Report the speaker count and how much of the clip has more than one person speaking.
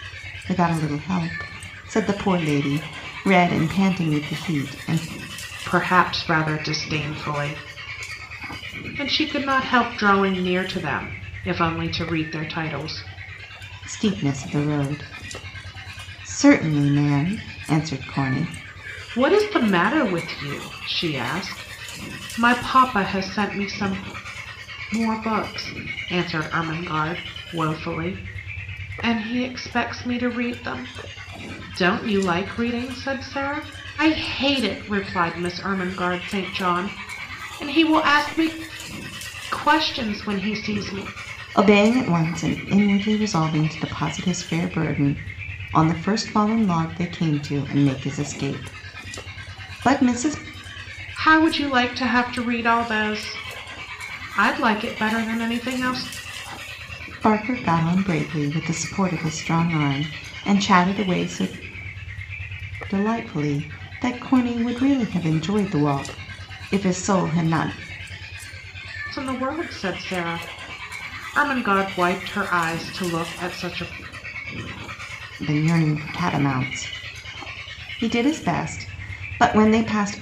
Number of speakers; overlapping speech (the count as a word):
two, no overlap